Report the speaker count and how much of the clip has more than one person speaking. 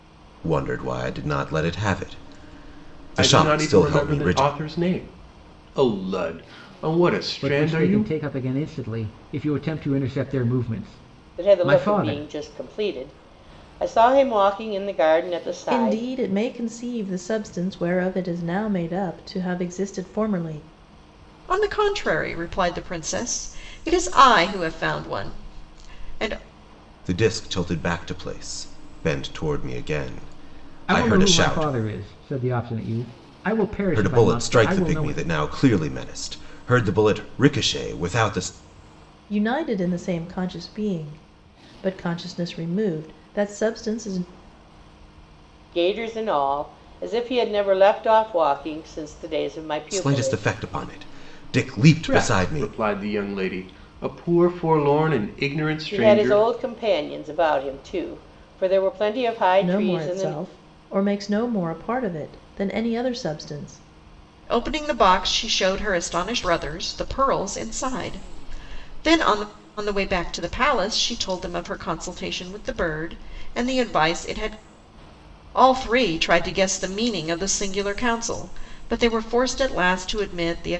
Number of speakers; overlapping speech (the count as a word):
six, about 11%